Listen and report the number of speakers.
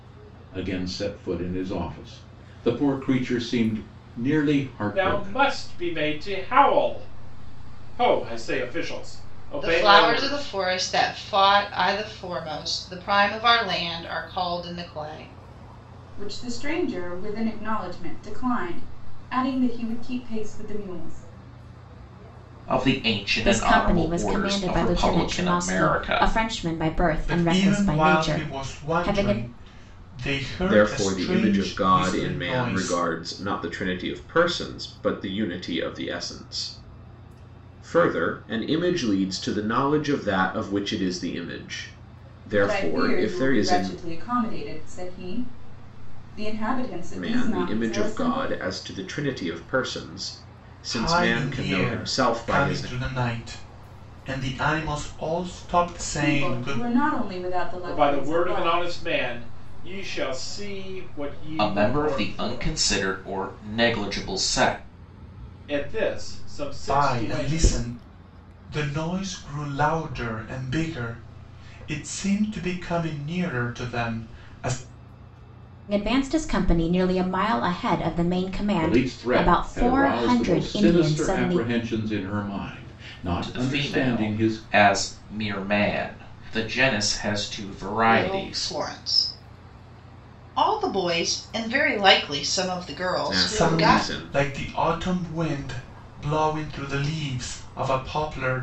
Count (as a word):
eight